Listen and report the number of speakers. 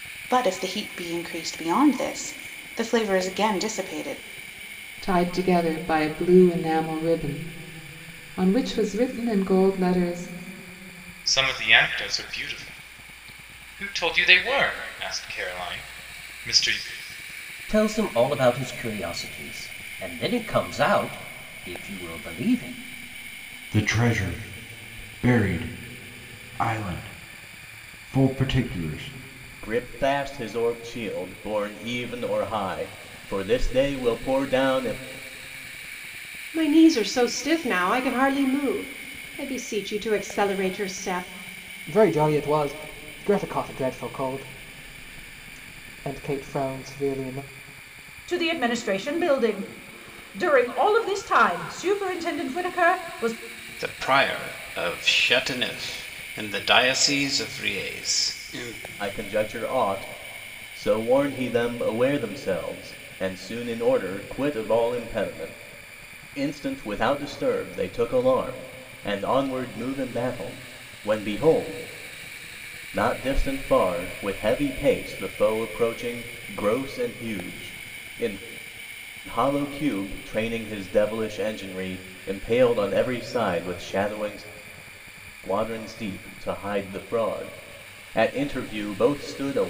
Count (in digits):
10